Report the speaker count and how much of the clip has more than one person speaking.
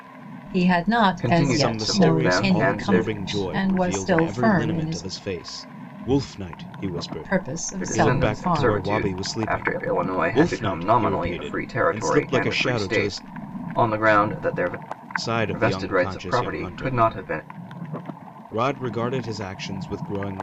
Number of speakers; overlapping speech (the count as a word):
three, about 56%